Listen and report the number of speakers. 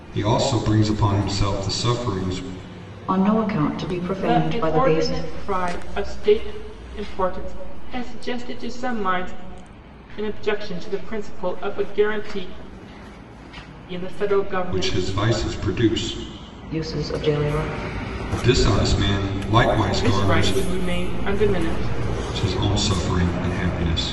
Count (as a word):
three